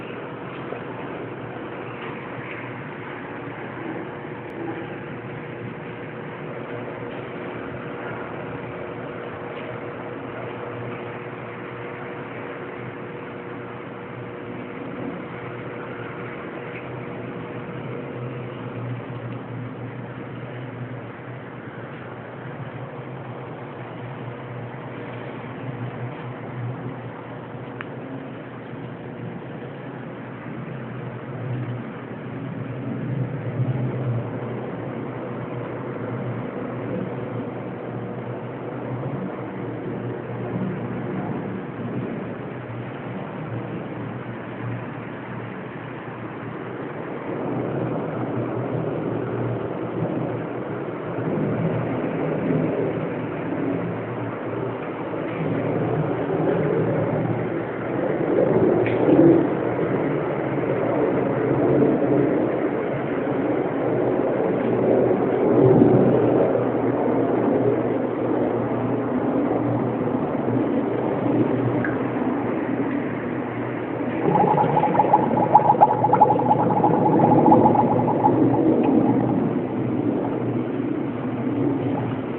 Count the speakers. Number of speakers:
0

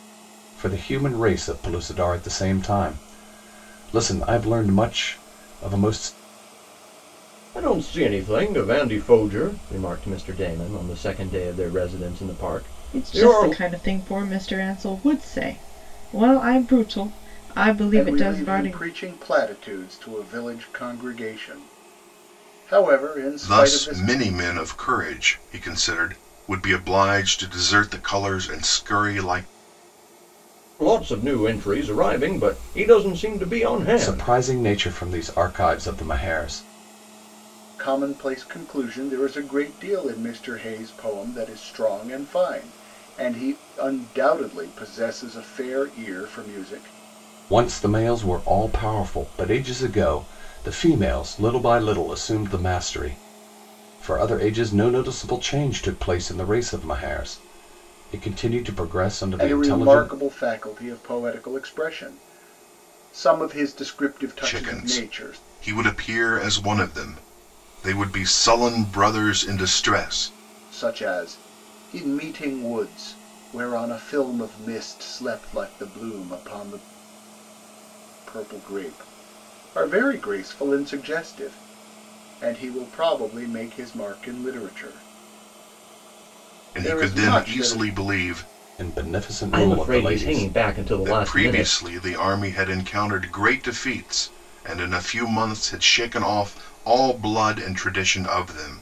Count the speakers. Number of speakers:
5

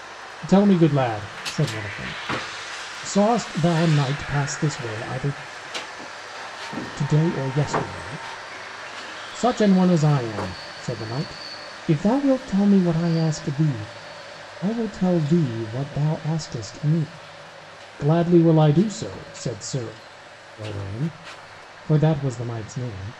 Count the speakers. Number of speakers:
1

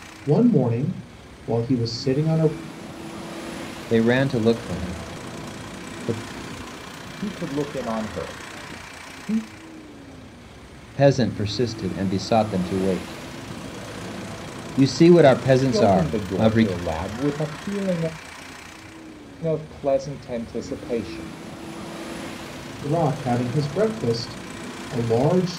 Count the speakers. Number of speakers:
3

